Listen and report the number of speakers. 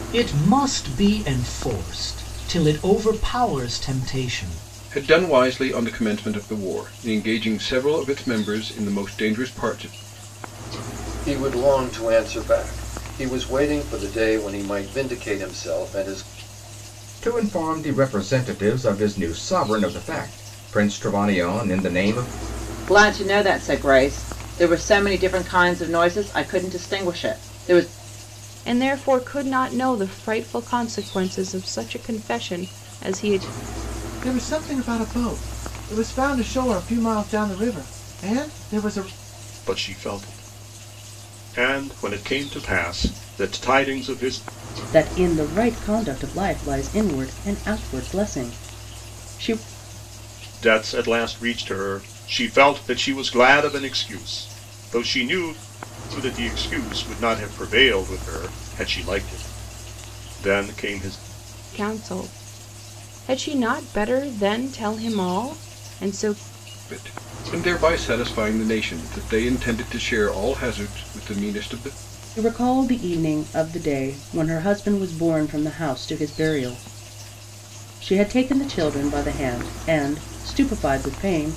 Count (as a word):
nine